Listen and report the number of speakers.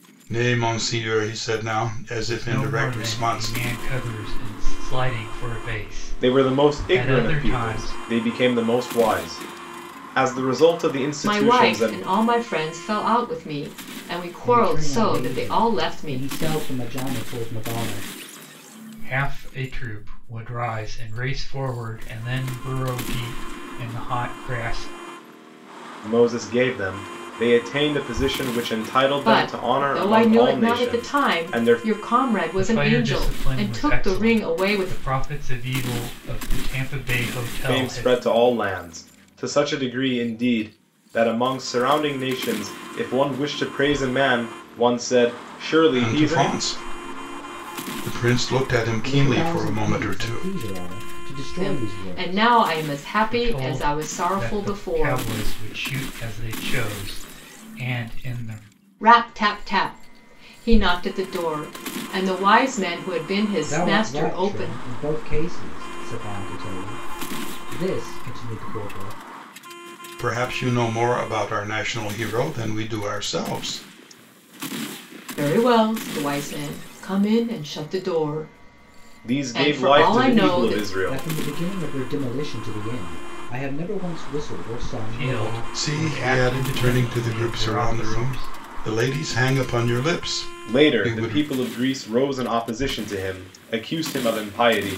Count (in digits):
5